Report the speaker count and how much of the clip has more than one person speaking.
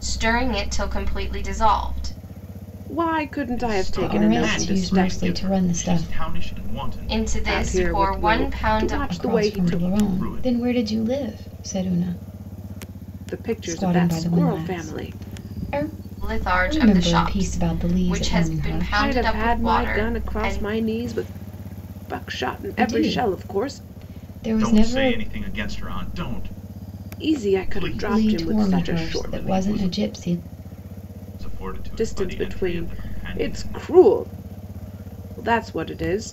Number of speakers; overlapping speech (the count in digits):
4, about 48%